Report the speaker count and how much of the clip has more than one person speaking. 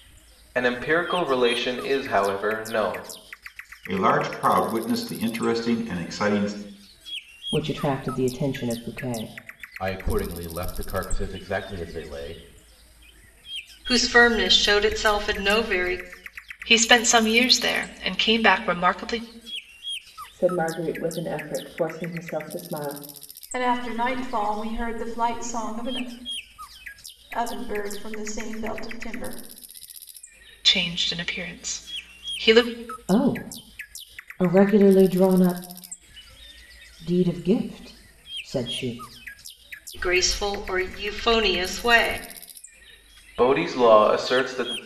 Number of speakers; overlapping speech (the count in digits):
8, no overlap